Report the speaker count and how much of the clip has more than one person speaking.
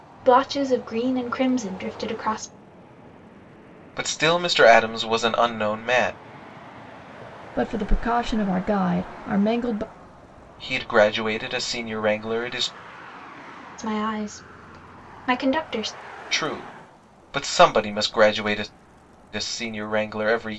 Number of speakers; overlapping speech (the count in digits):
3, no overlap